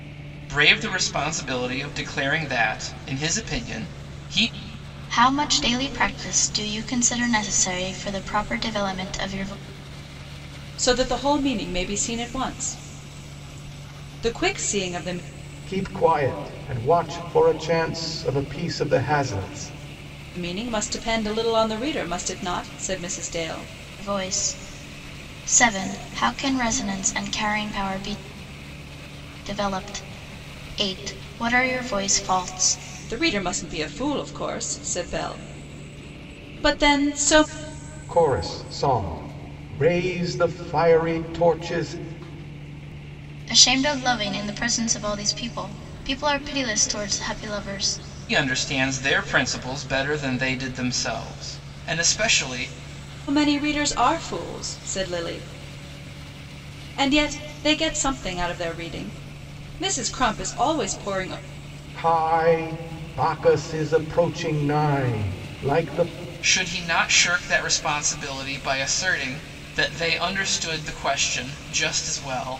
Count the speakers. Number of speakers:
4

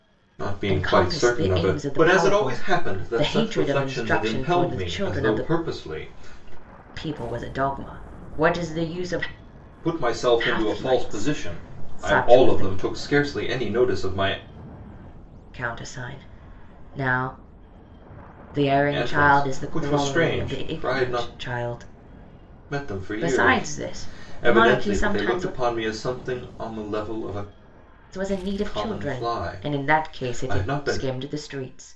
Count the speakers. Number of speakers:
2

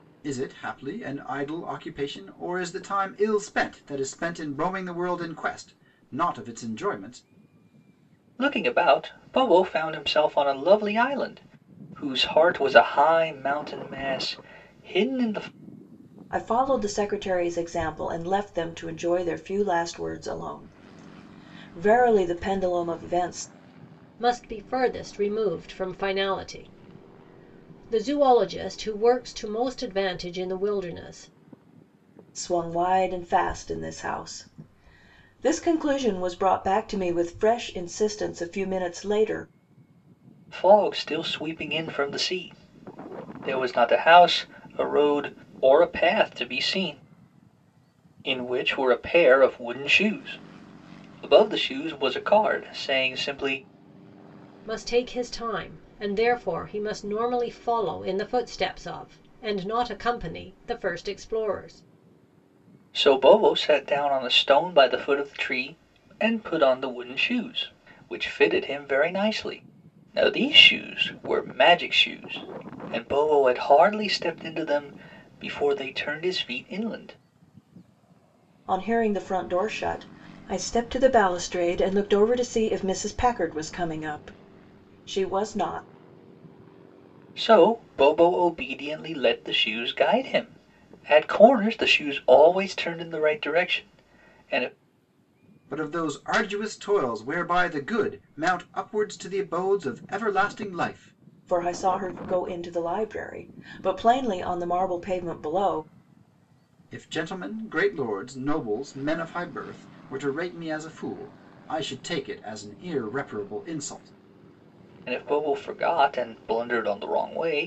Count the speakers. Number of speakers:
4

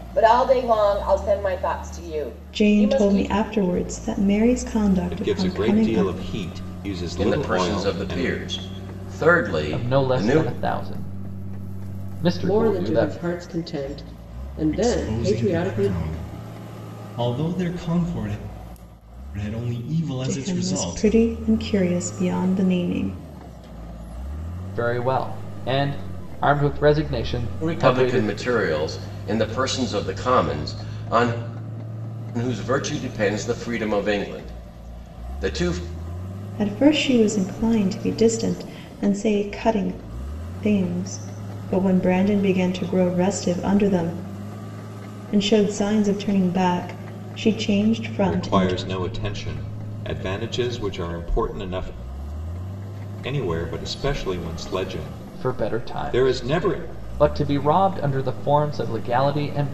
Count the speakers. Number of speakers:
7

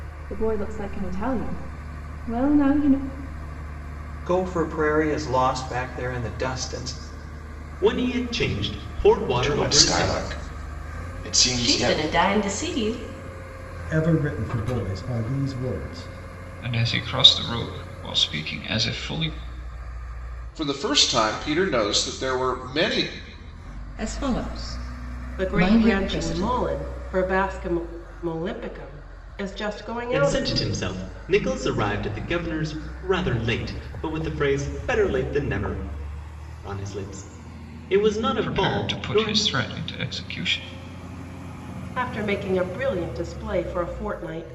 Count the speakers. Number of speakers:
10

